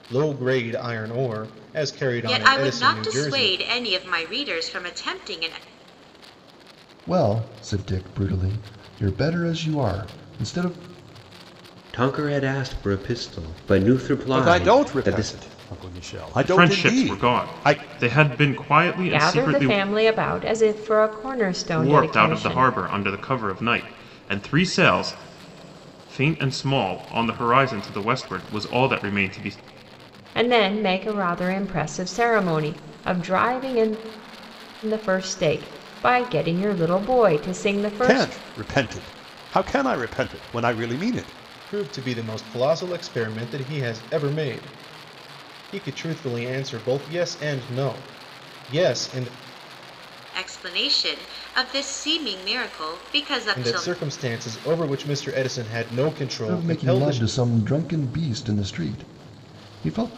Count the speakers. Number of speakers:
7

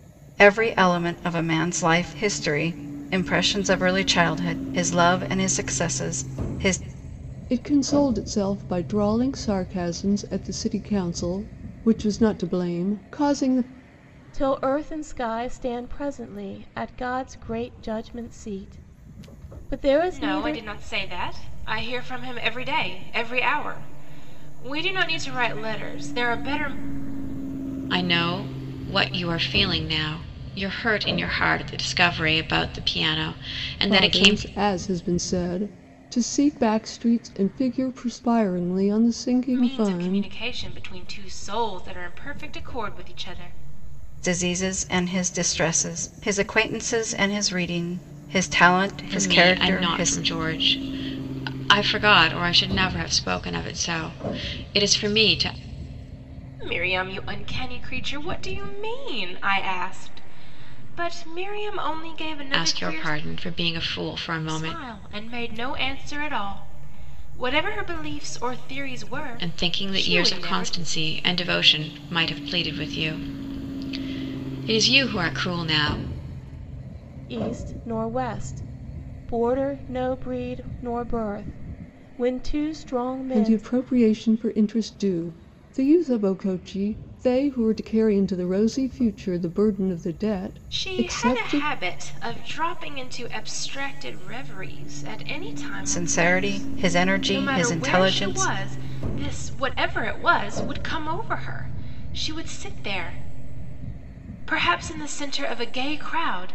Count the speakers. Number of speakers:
5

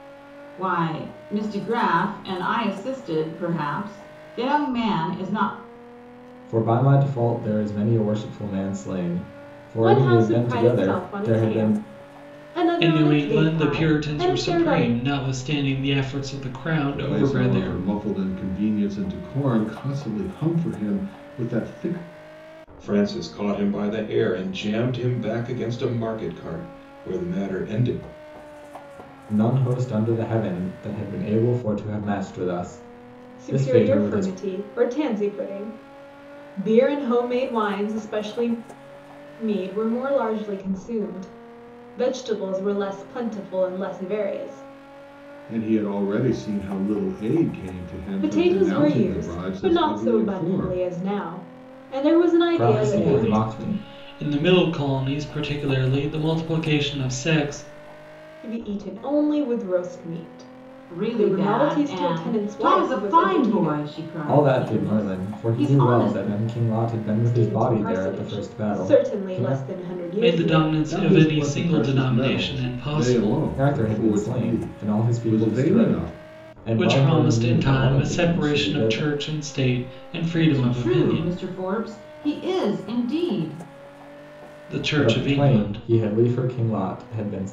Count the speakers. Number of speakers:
6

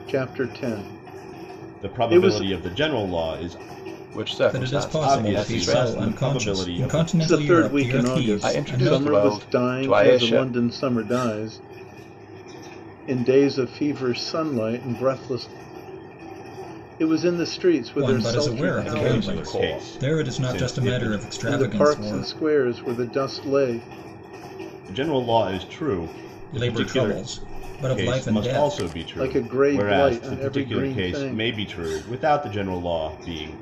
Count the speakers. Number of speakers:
4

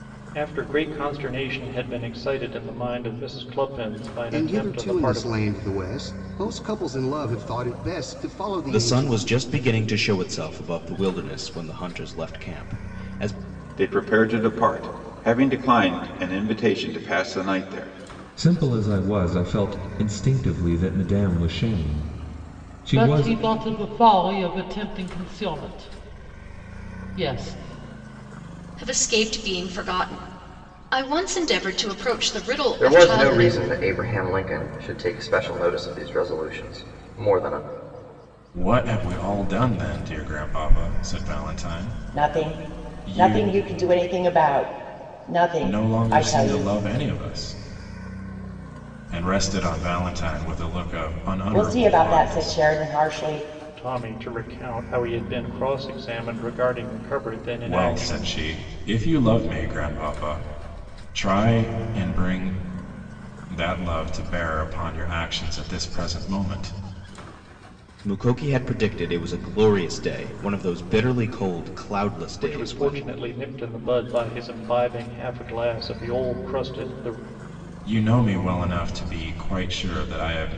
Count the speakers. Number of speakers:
10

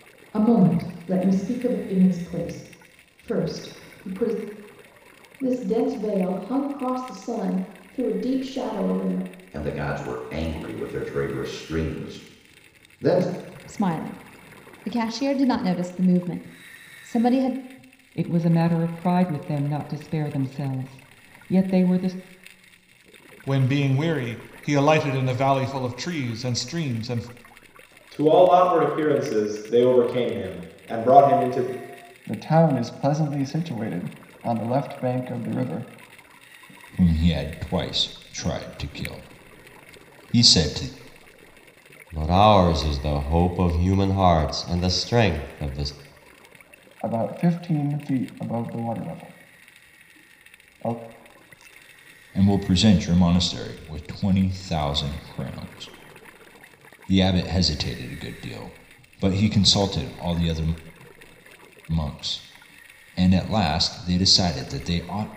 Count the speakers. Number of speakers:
10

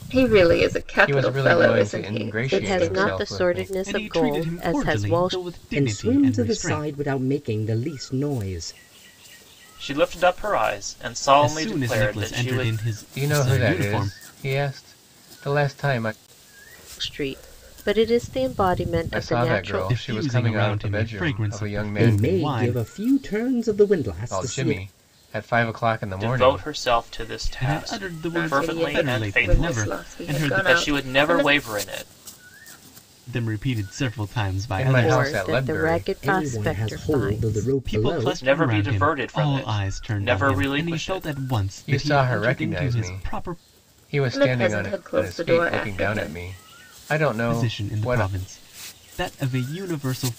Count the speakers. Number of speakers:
6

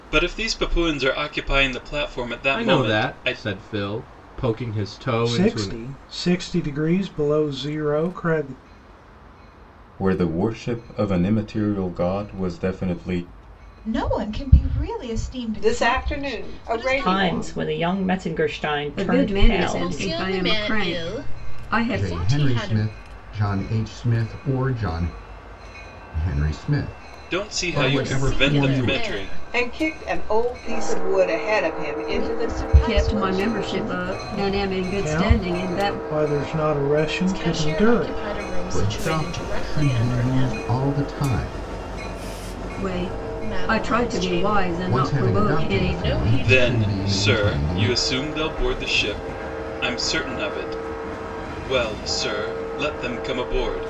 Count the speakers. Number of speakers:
10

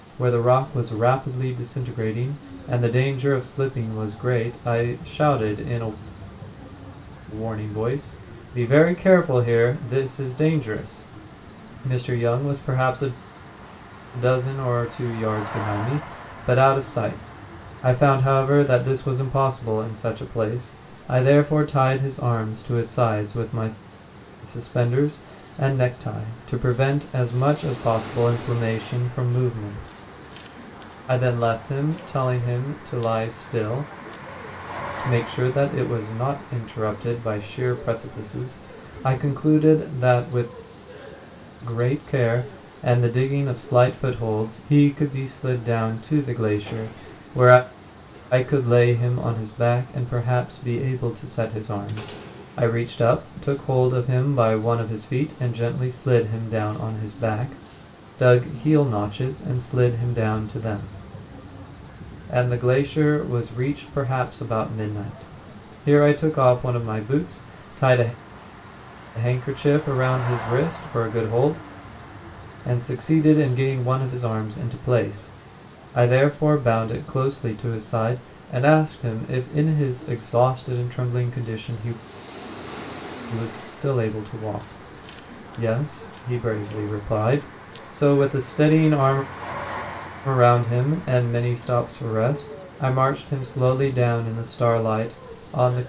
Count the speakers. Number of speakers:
1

